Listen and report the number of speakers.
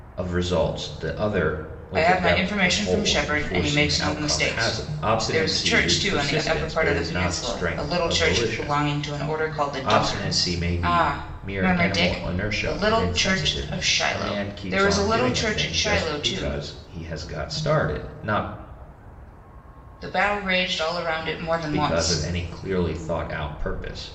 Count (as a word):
two